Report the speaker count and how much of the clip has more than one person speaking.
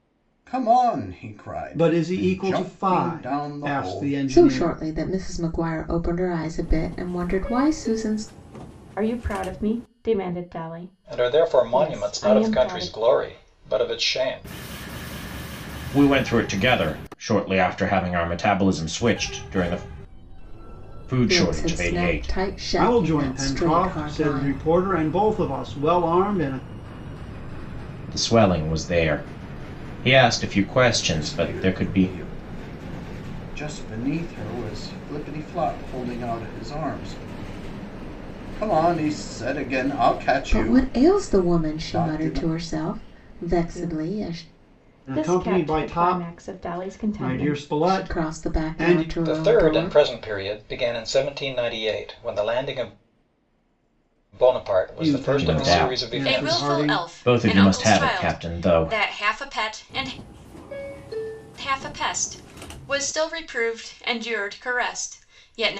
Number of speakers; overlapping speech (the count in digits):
6, about 31%